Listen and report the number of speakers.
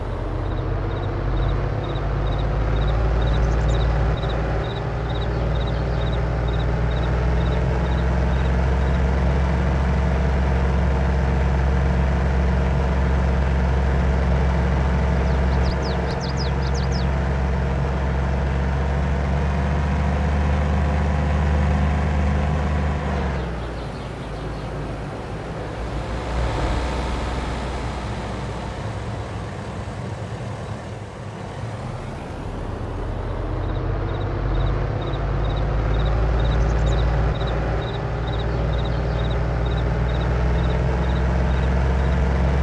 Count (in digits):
0